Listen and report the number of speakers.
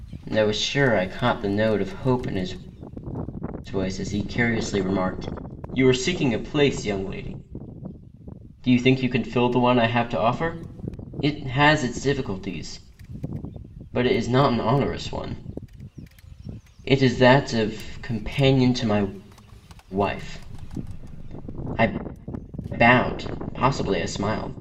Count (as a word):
one